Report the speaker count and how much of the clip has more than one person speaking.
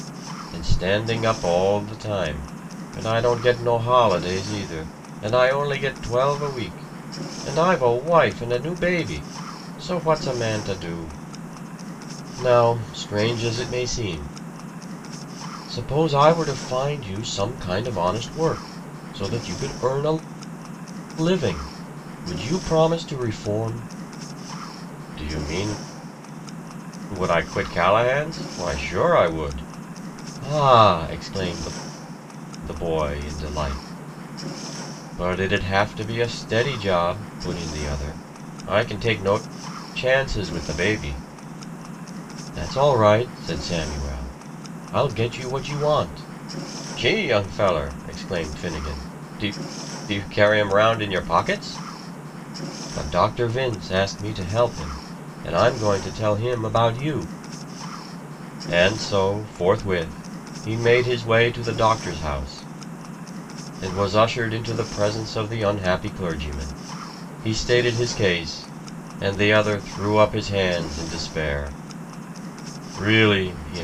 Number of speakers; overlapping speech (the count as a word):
one, no overlap